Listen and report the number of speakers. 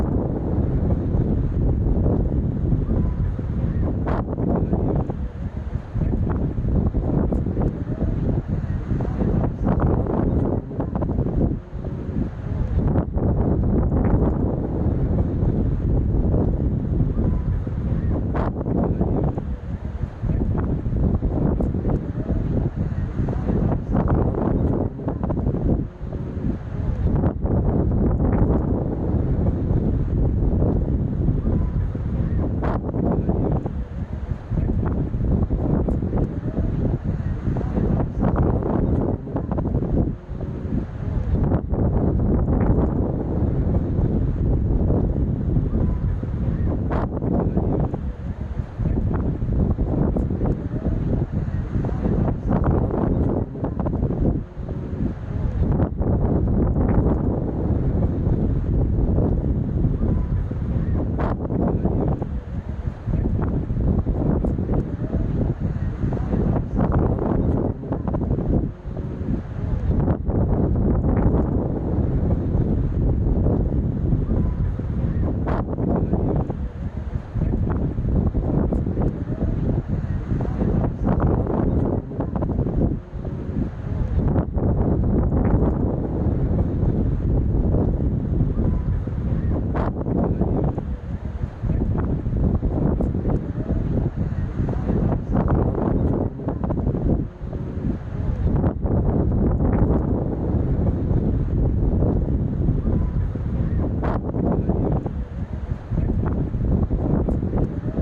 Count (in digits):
0